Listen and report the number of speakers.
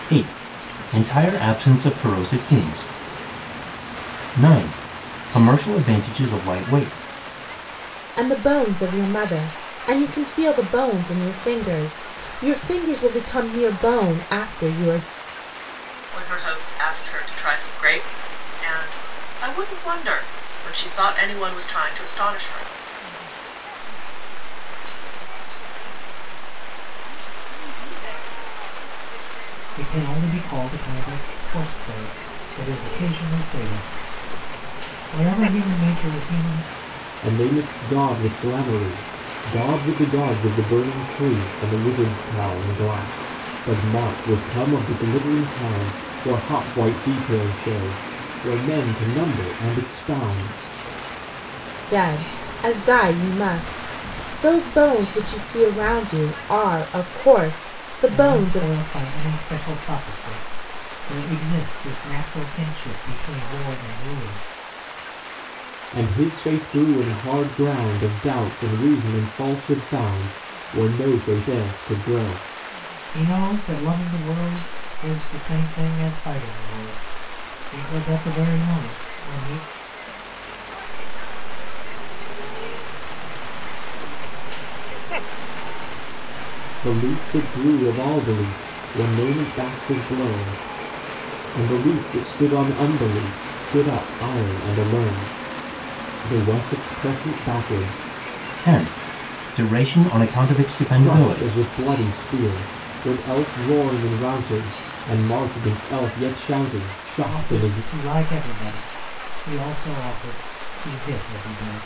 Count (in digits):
6